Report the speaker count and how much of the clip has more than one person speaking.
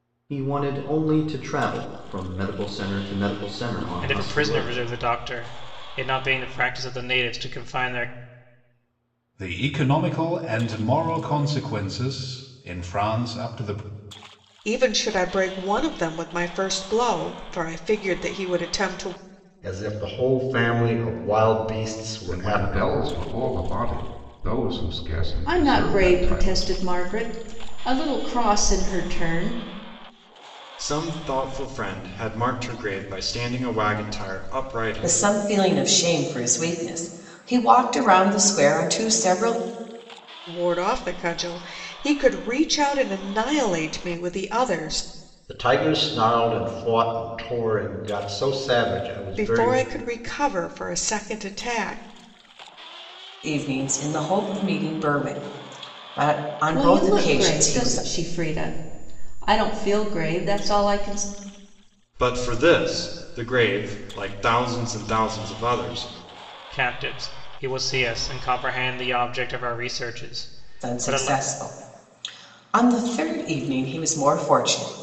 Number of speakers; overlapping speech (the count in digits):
9, about 8%